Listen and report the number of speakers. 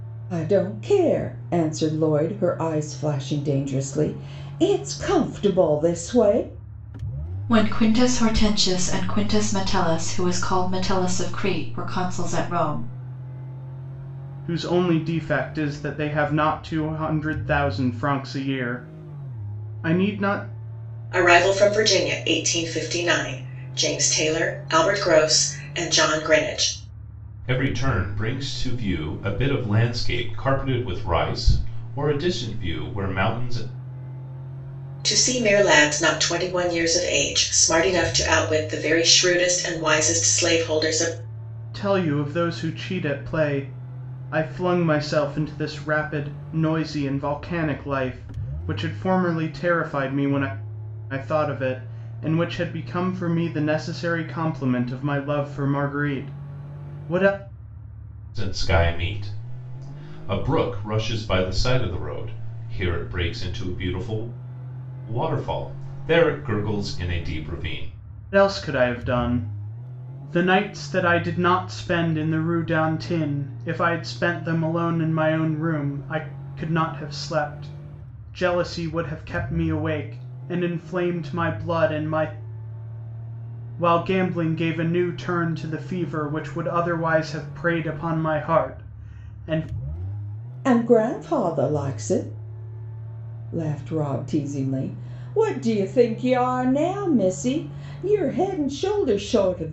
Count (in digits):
5